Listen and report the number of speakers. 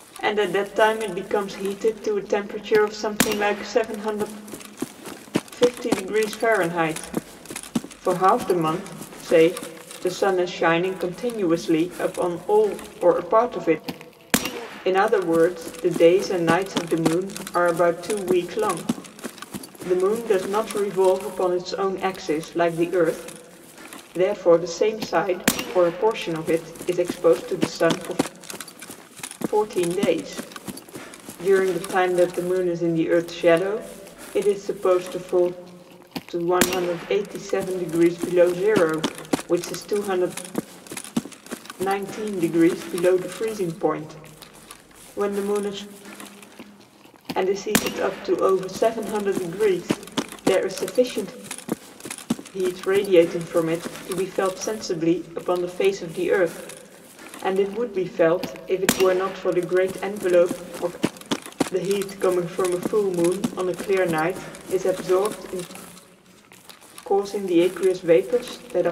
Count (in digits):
1